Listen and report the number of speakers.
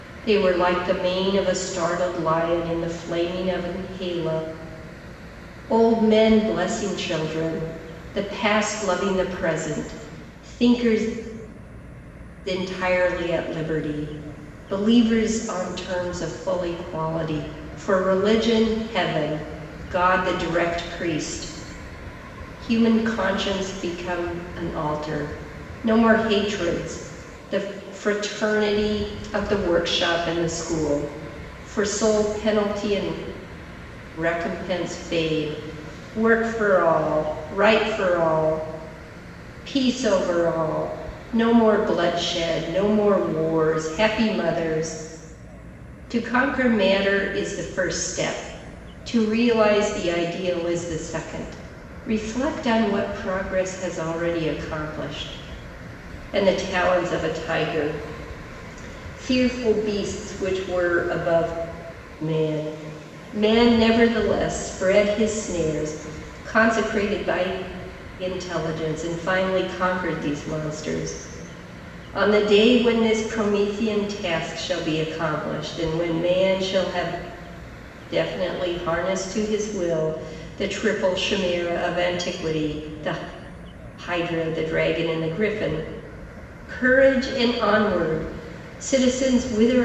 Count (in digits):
1